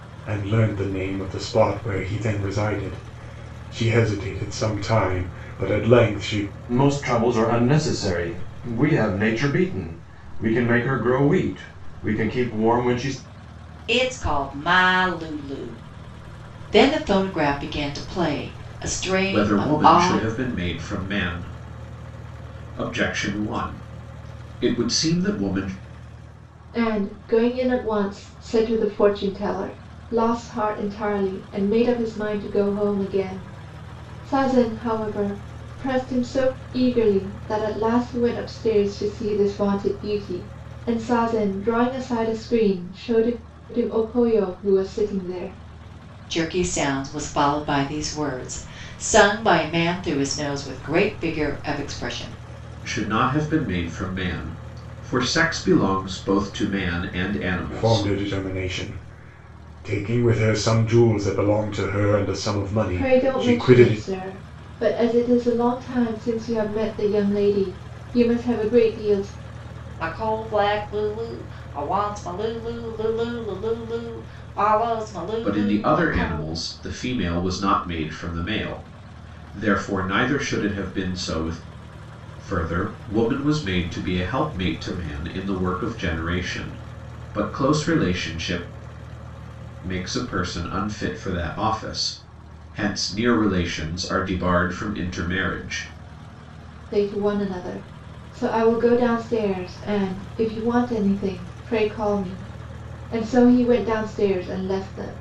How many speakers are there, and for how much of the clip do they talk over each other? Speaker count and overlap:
5, about 3%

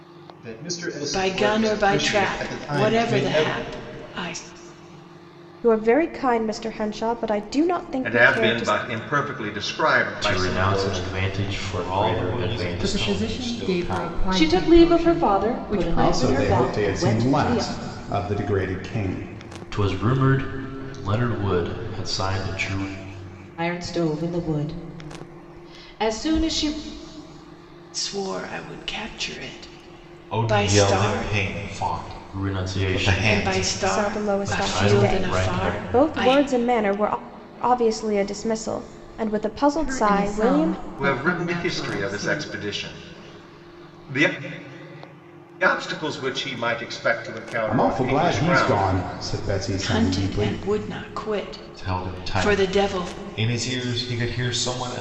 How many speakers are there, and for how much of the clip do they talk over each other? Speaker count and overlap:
9, about 39%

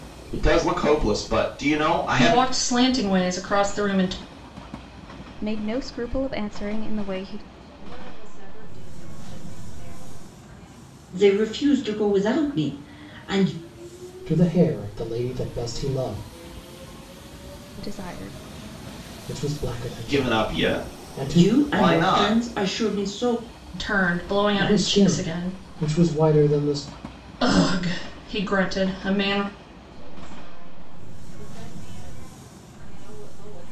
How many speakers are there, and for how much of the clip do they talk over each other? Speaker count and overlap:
6, about 11%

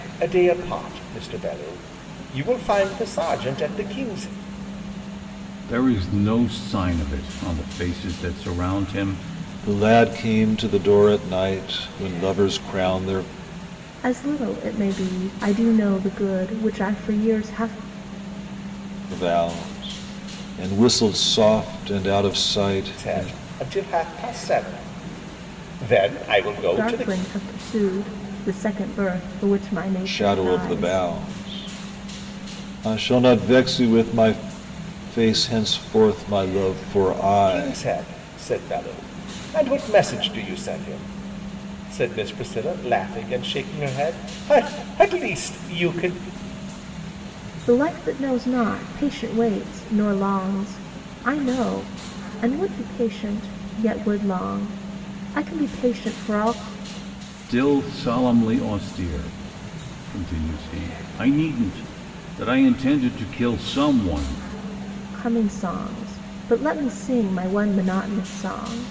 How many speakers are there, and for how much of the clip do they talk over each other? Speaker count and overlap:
4, about 3%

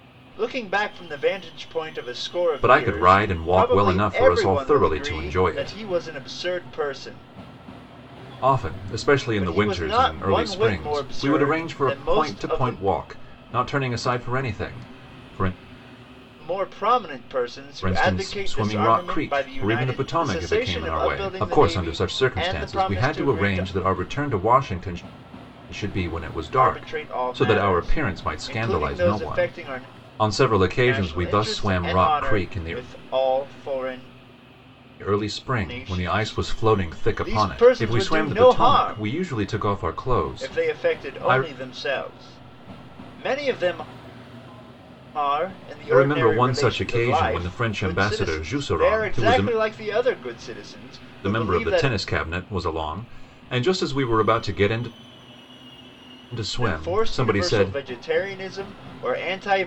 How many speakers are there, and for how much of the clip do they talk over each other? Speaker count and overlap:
2, about 47%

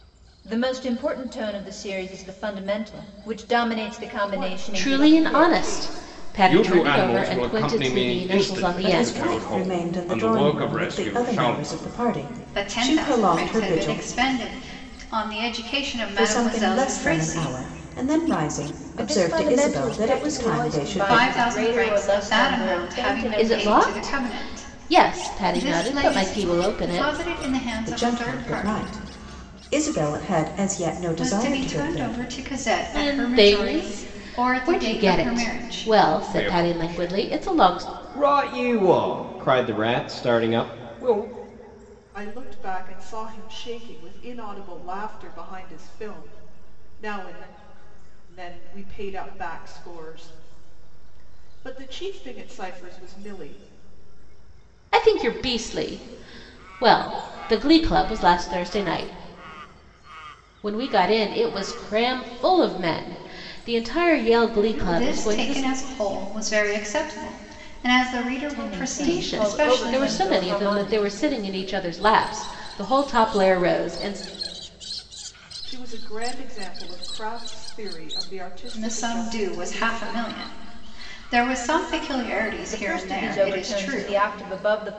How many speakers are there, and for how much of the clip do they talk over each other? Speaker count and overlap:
6, about 38%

